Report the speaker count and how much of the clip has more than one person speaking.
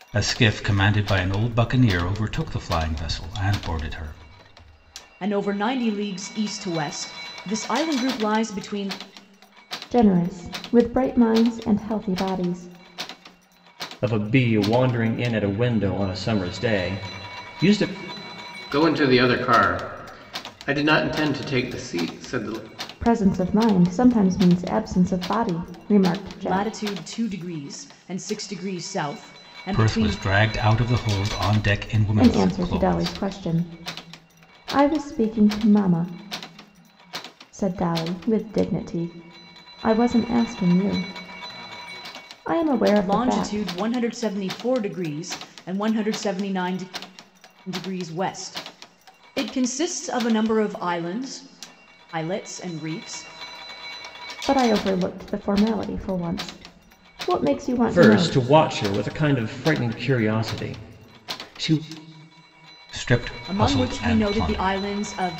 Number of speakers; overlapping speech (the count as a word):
five, about 7%